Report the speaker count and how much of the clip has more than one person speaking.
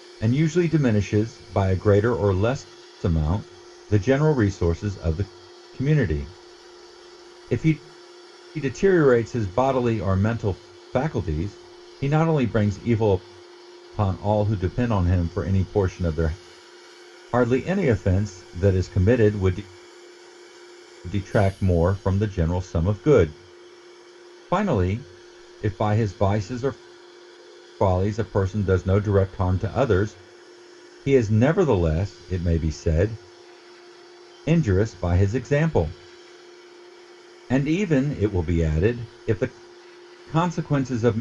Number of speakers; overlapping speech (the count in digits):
1, no overlap